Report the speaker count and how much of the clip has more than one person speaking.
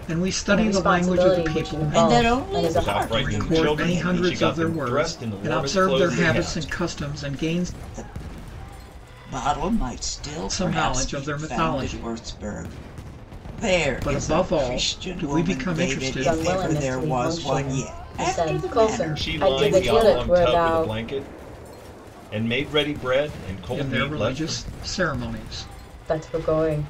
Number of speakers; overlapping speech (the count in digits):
4, about 61%